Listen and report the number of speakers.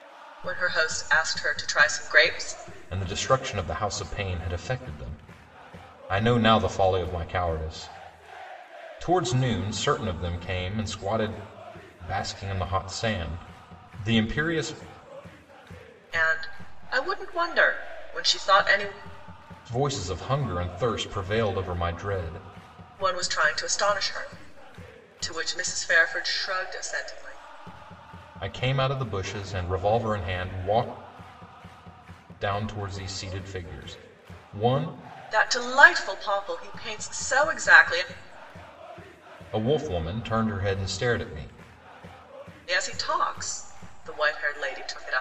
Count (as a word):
two